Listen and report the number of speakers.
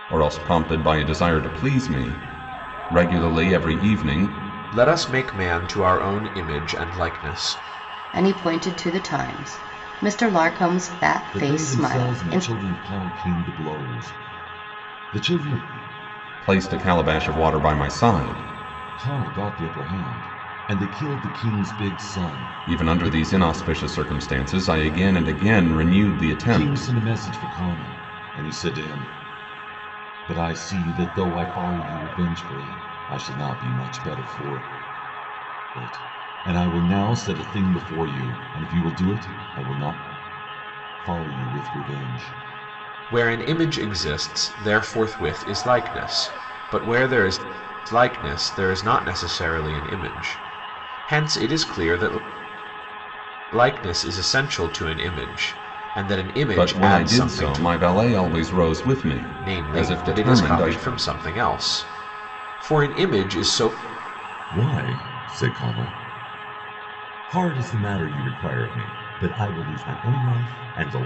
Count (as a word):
four